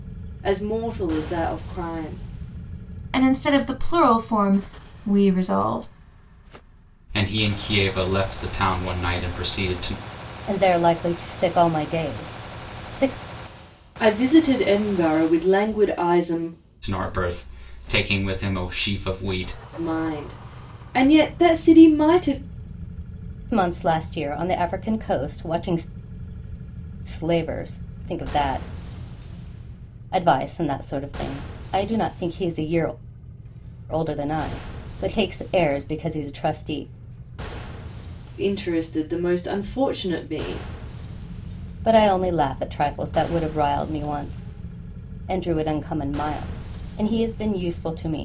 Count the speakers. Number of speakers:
4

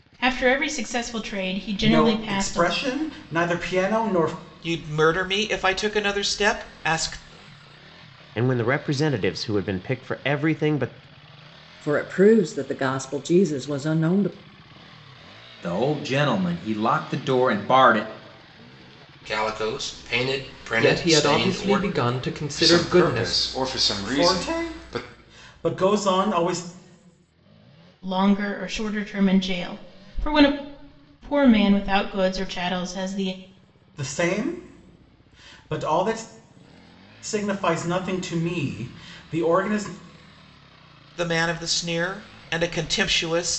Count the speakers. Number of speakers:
9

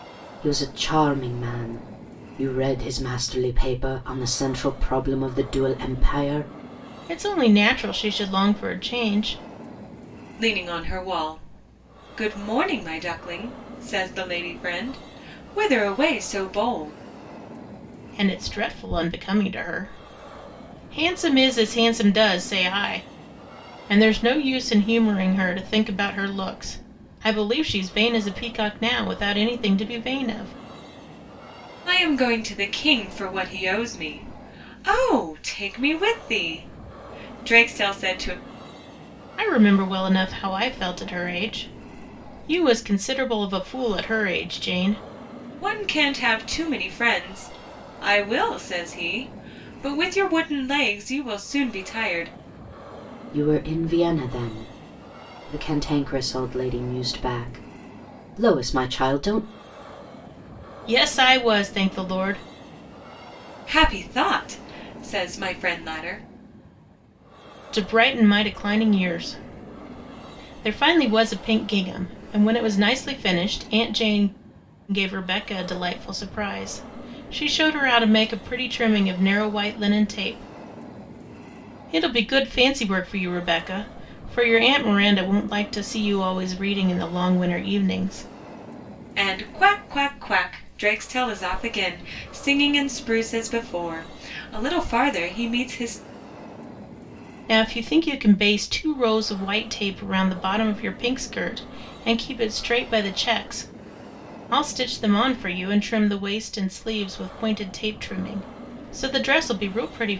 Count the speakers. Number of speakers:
3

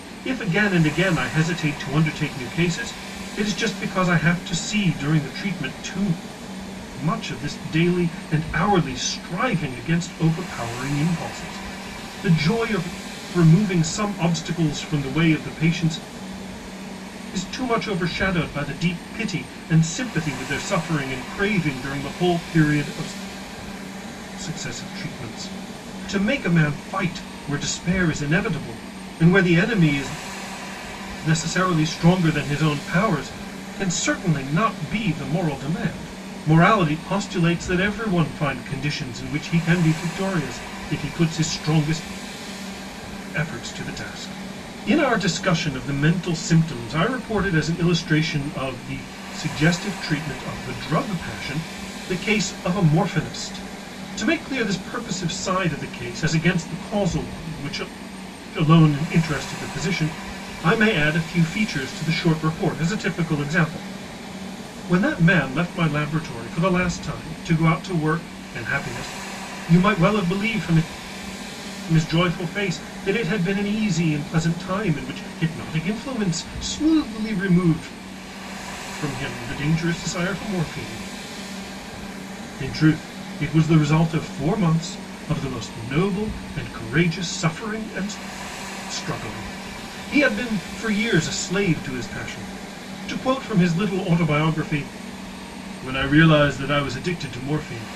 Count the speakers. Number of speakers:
1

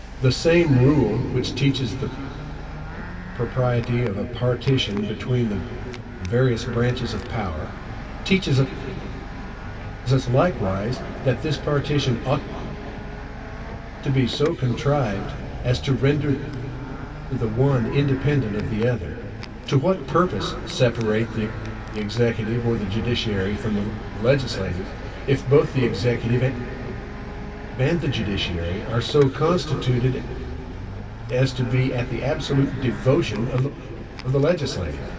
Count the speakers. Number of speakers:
1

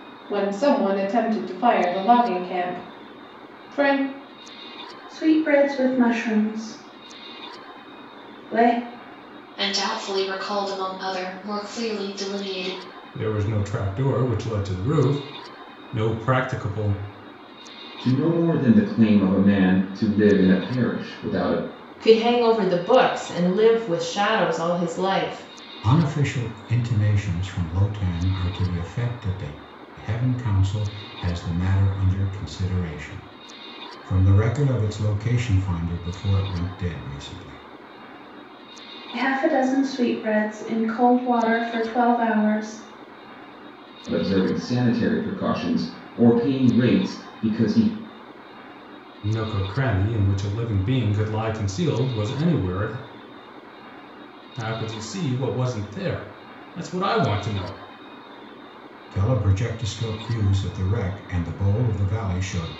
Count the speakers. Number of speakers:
7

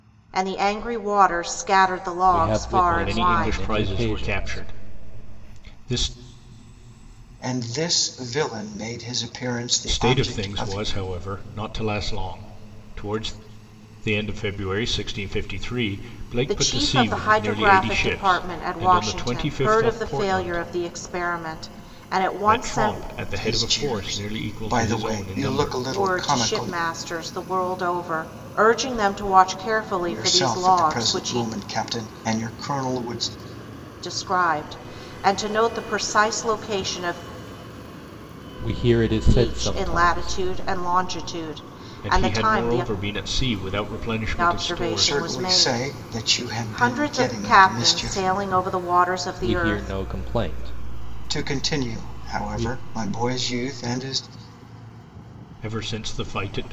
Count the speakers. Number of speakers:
4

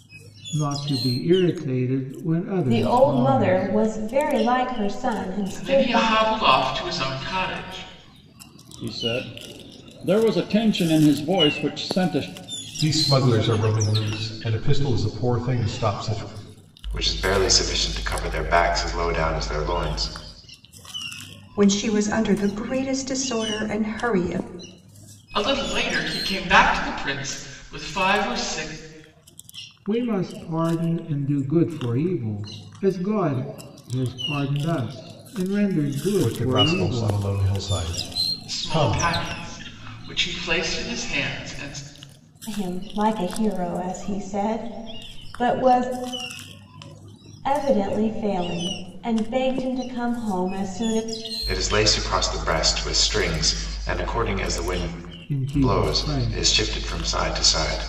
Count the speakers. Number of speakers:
7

